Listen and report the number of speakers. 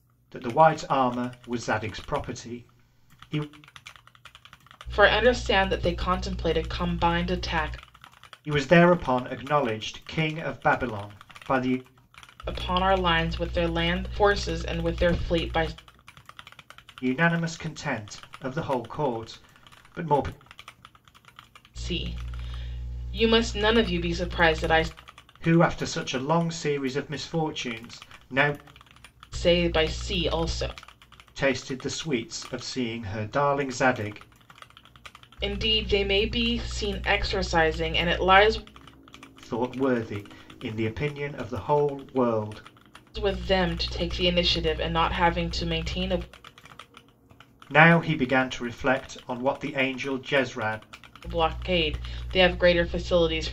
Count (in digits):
2